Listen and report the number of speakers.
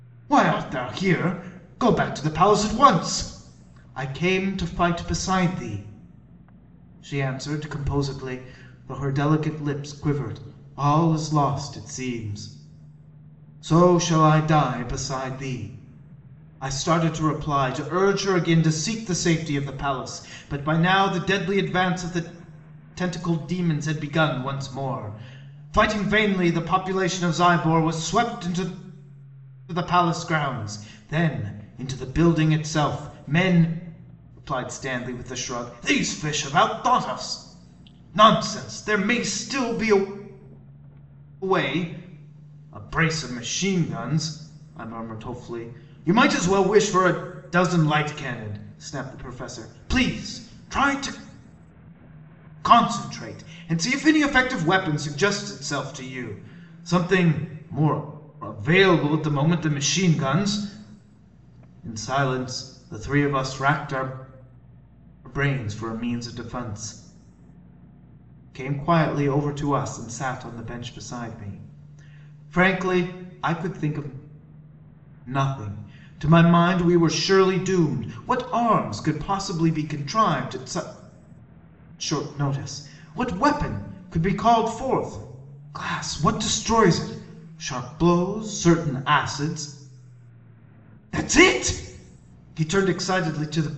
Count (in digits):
1